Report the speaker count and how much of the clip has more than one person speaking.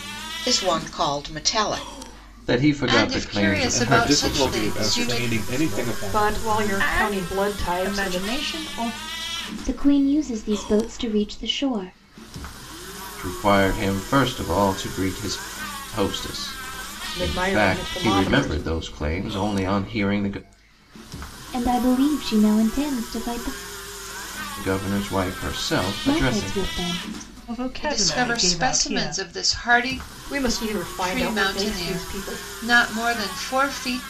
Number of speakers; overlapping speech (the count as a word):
eight, about 31%